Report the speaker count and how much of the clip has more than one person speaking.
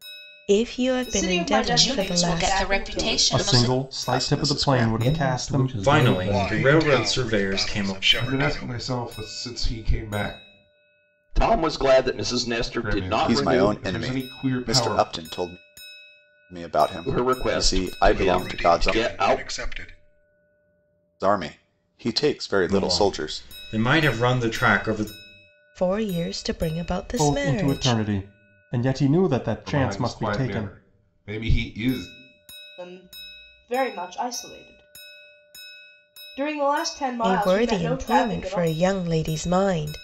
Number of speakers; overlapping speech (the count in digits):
10, about 41%